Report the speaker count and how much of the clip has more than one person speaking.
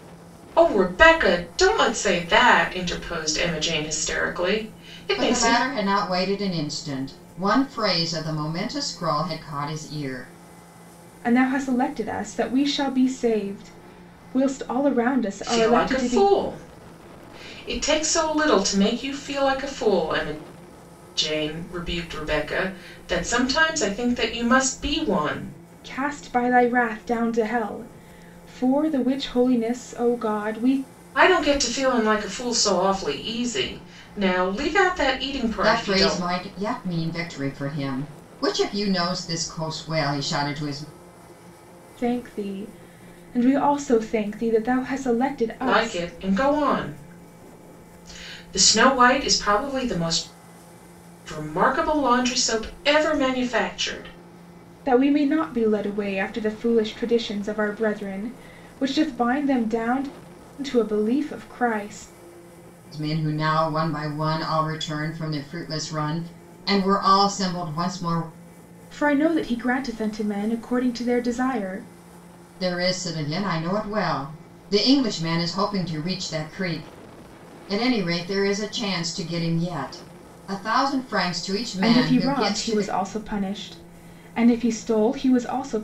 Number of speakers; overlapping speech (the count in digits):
3, about 4%